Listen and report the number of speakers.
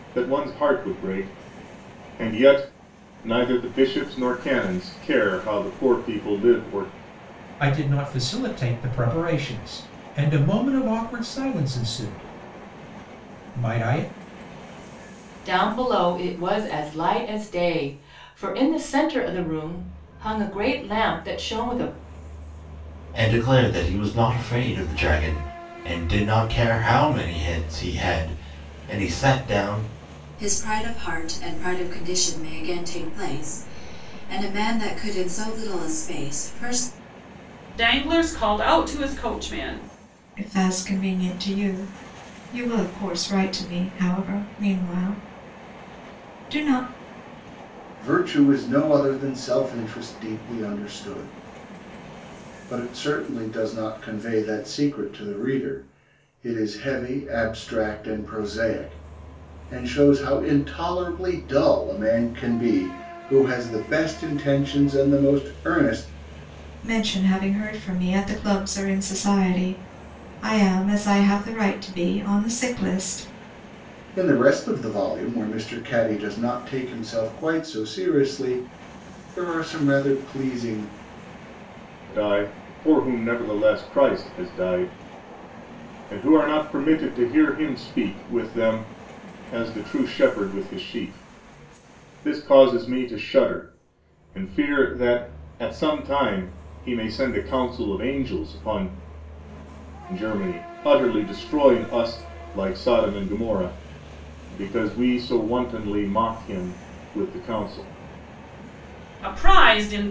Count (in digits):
8